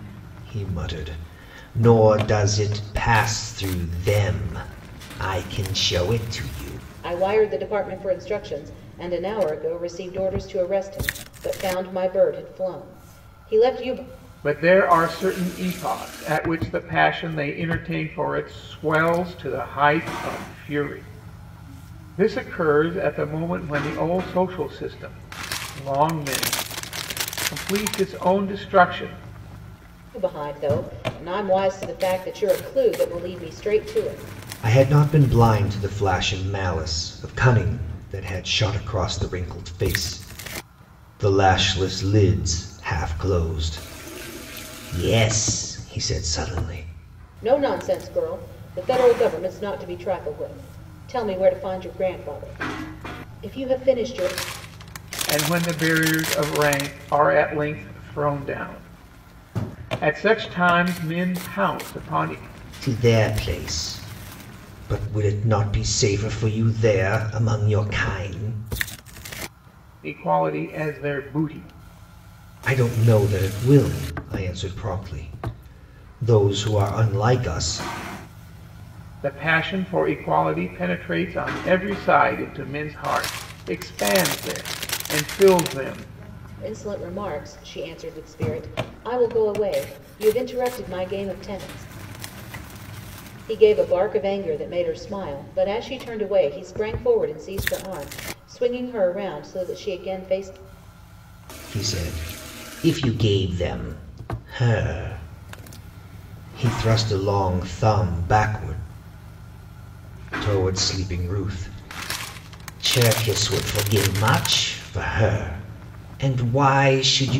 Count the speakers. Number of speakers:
three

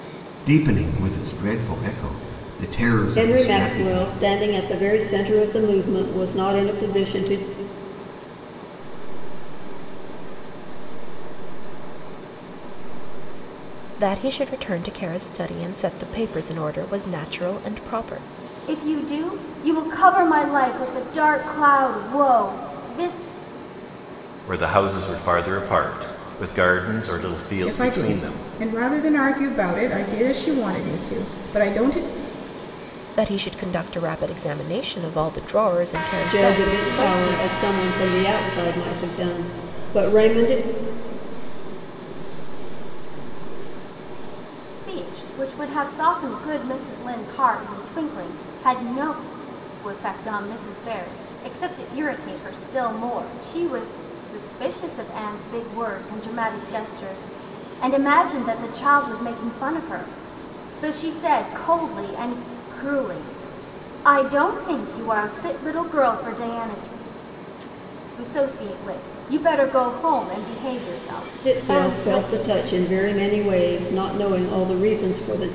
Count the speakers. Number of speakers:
seven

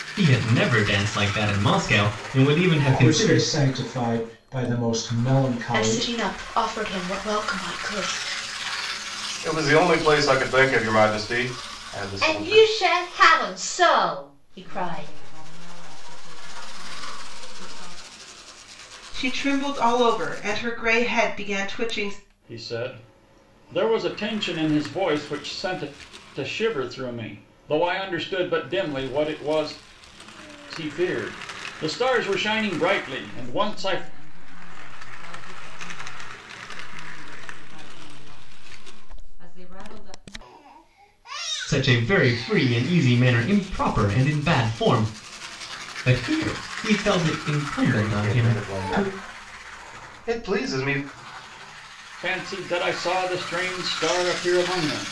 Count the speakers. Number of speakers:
eight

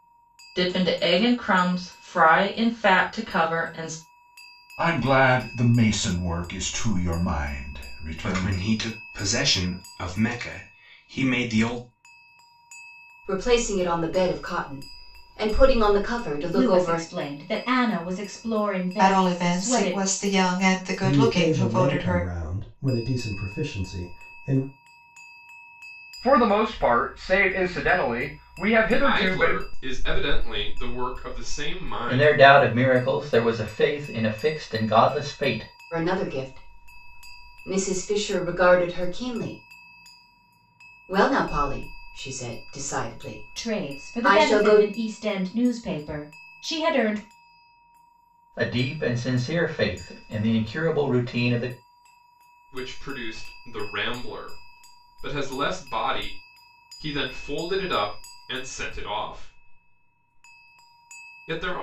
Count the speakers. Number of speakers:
ten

